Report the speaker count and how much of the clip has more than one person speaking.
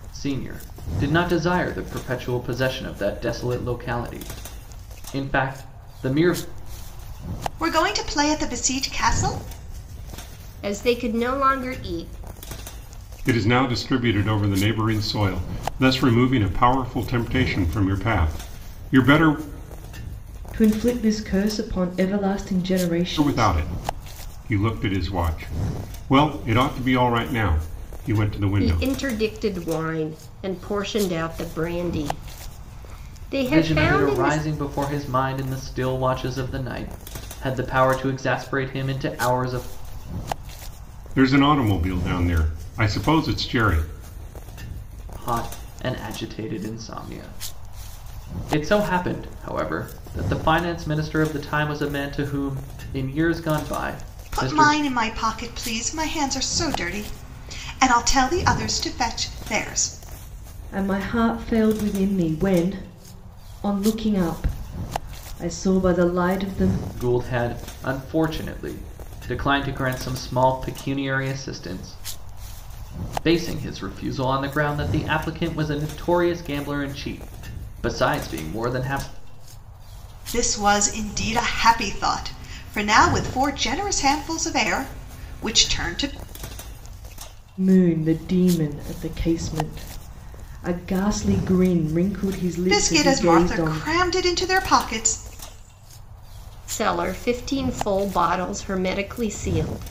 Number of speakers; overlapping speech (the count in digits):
5, about 3%